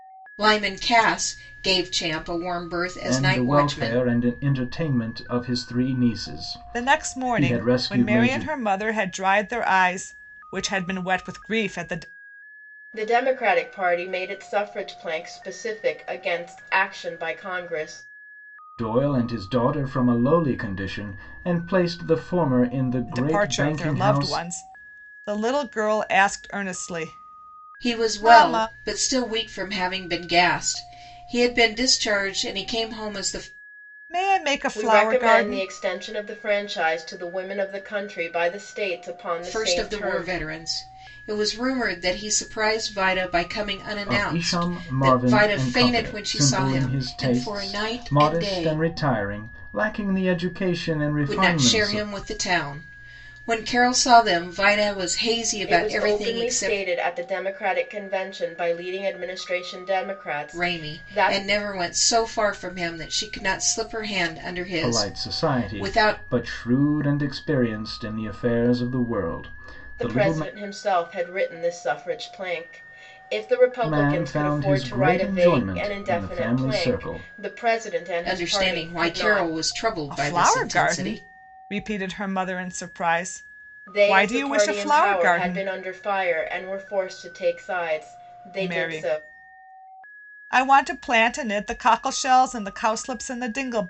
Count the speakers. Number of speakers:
four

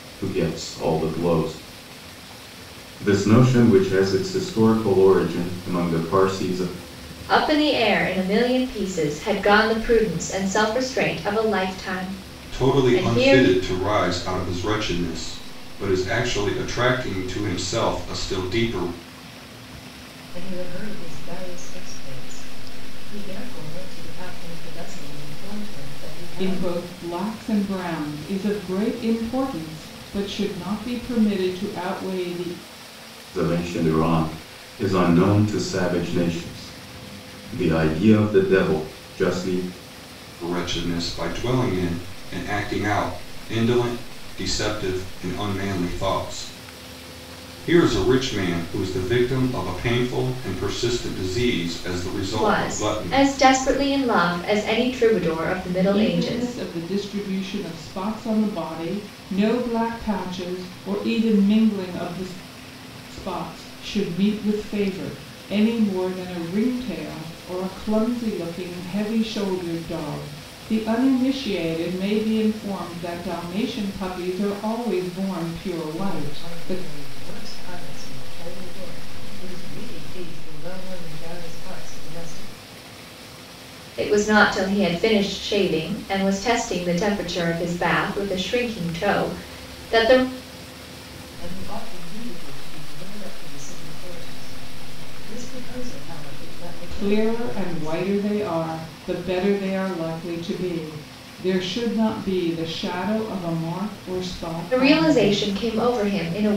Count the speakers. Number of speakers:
five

